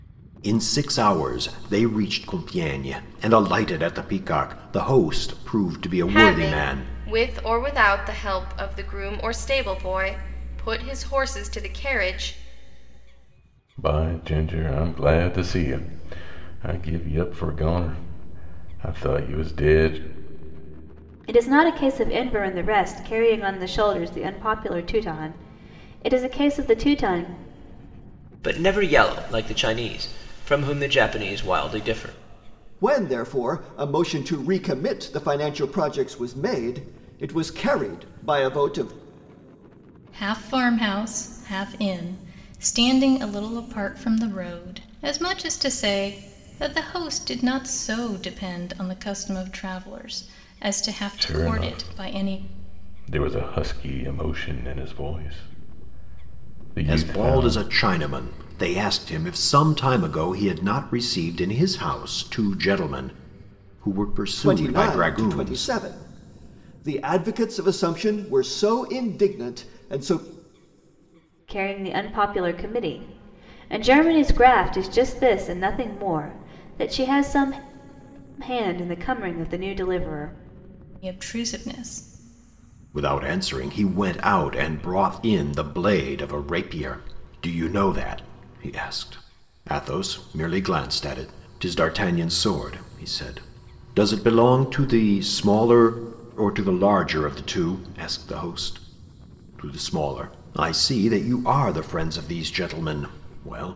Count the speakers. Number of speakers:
7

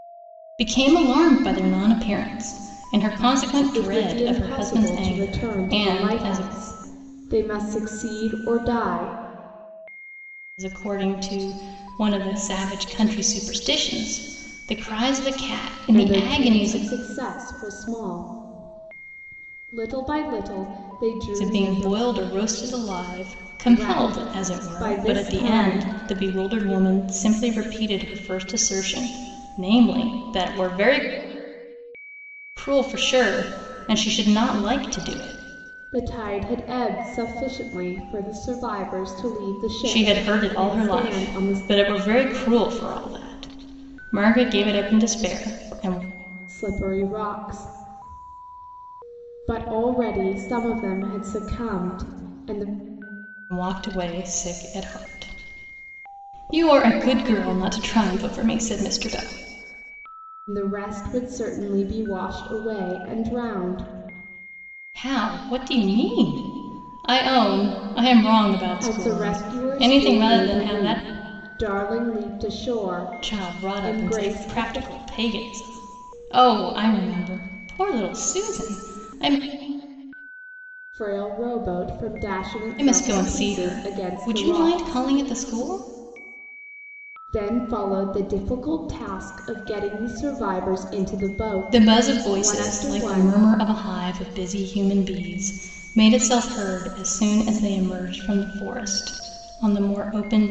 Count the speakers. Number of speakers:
2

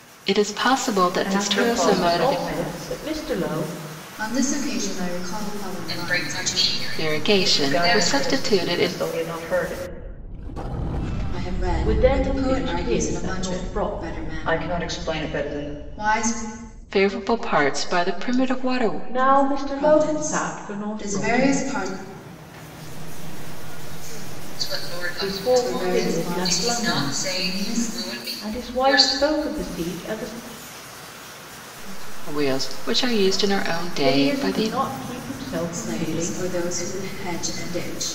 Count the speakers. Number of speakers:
6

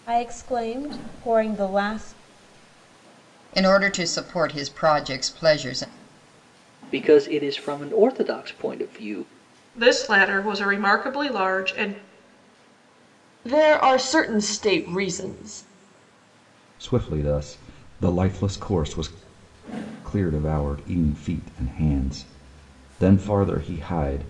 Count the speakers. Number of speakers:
6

